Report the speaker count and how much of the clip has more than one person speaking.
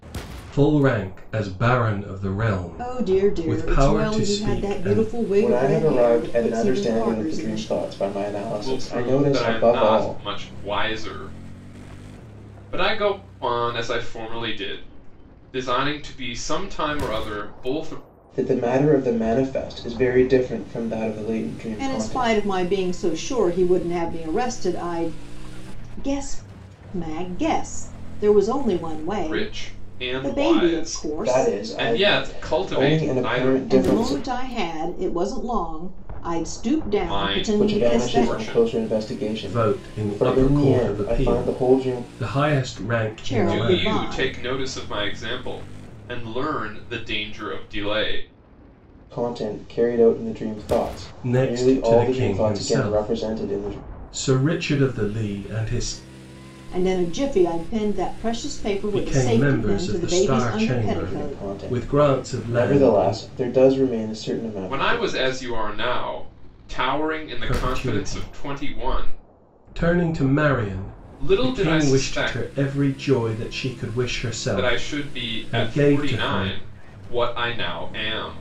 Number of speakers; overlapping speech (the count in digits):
4, about 39%